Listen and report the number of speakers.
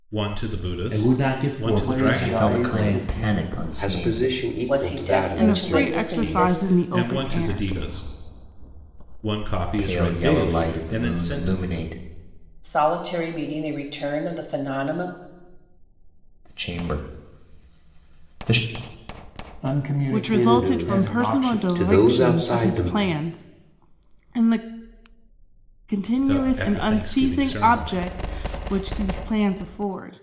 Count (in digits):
7